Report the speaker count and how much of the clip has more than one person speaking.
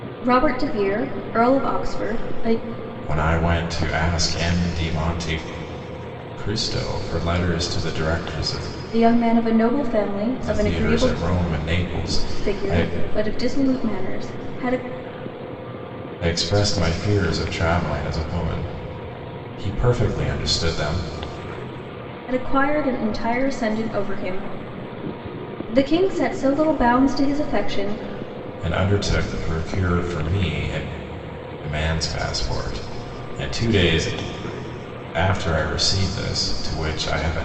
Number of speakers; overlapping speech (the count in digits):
2, about 4%